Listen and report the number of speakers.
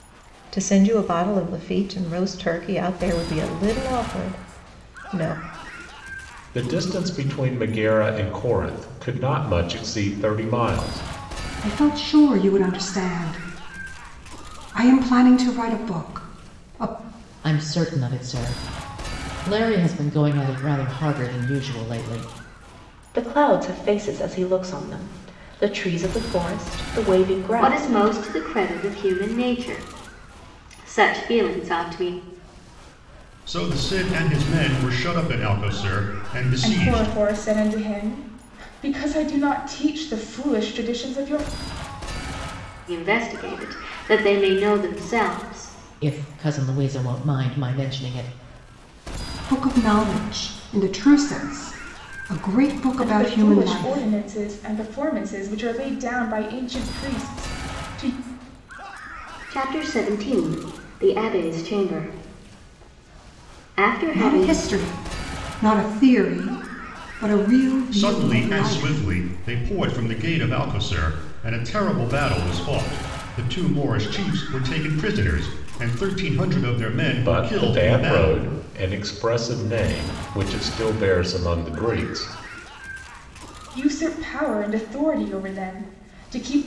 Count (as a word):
eight